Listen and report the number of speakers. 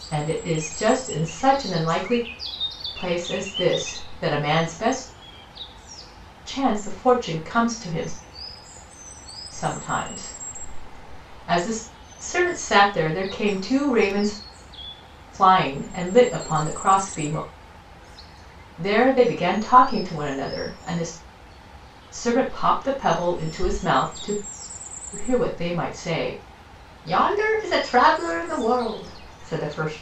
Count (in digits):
1